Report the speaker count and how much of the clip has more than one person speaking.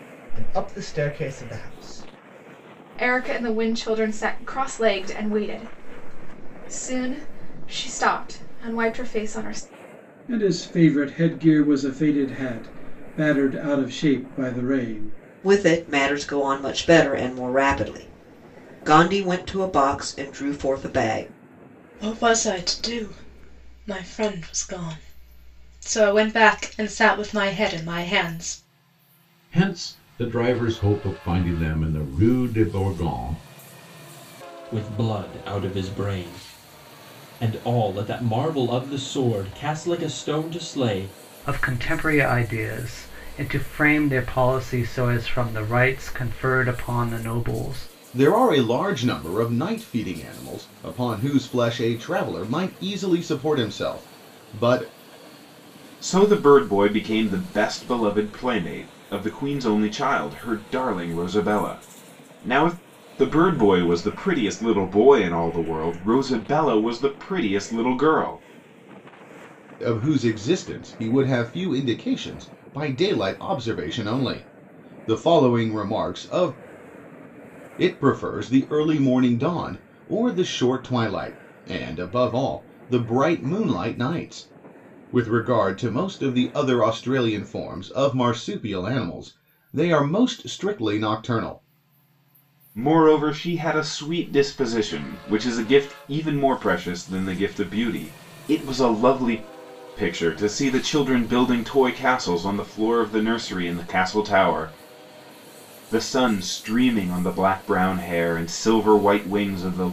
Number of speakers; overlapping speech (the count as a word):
ten, no overlap